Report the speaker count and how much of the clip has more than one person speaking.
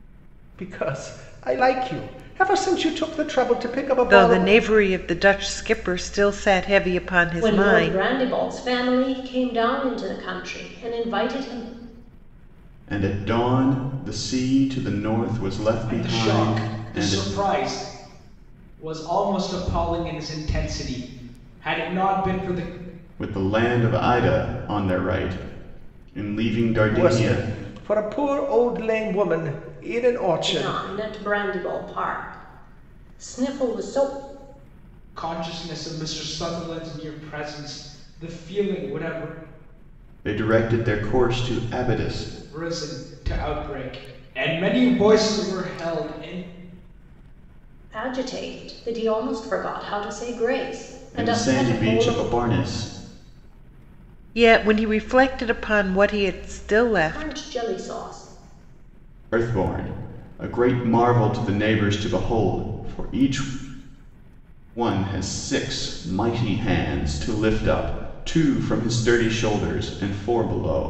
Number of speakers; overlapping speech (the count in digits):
5, about 7%